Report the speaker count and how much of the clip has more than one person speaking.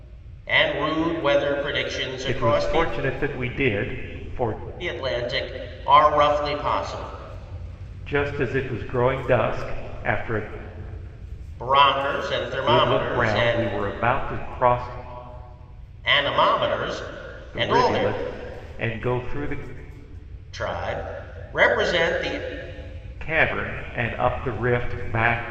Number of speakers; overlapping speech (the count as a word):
two, about 10%